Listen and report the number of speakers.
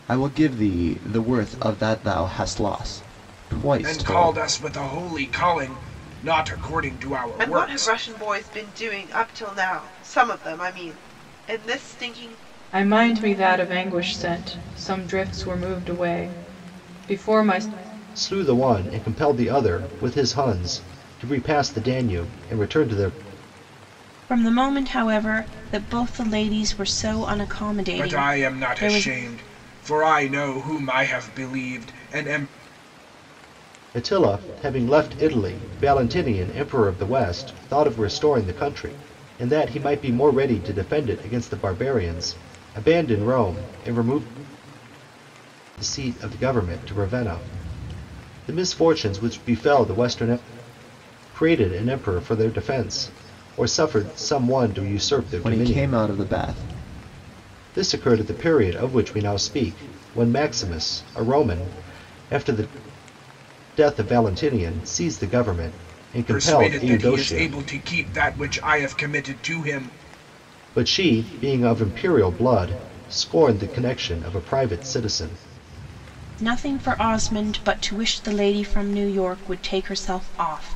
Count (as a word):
six